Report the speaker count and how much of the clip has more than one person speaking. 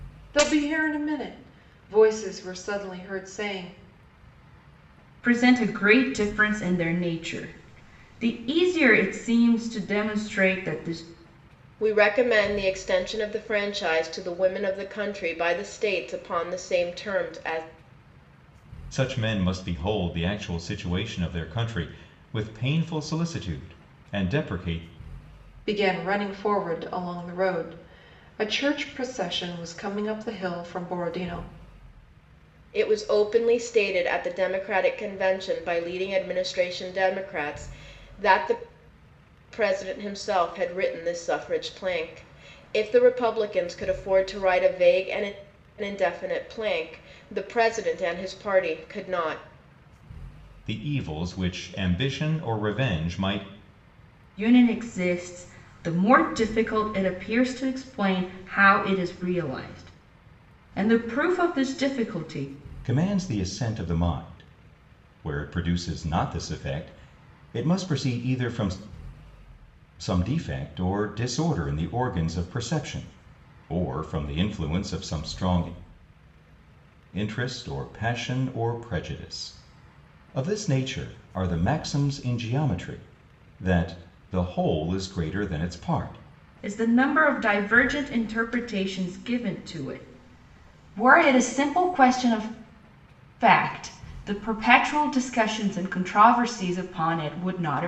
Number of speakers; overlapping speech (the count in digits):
4, no overlap